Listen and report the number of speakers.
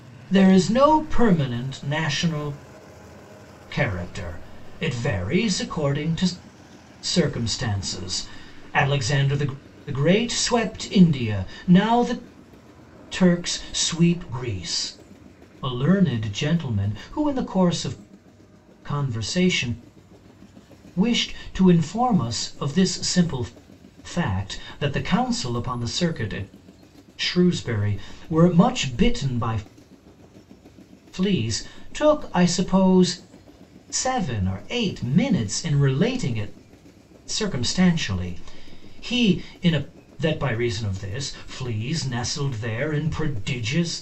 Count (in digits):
1